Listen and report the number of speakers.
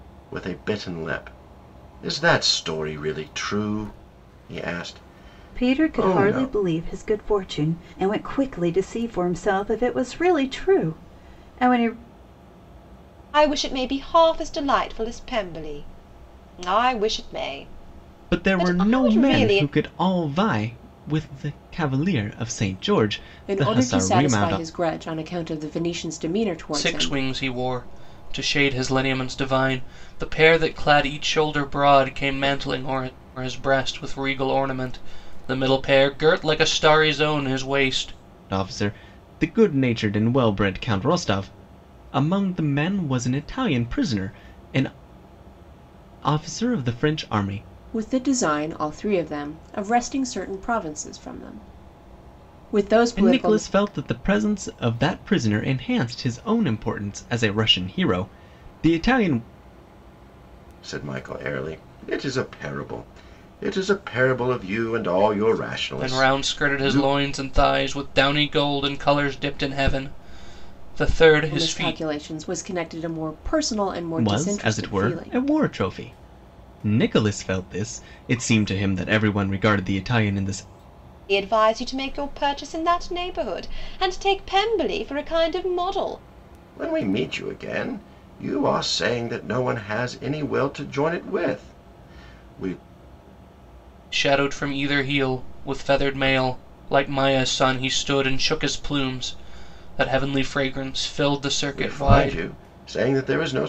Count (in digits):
6